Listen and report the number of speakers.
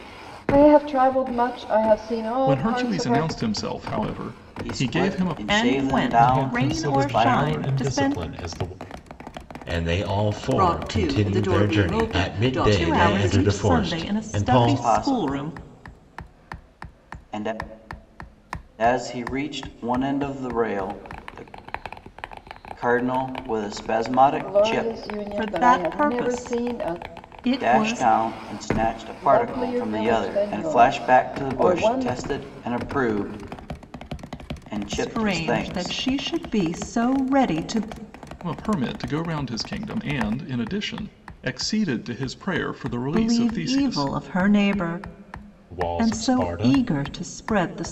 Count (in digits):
7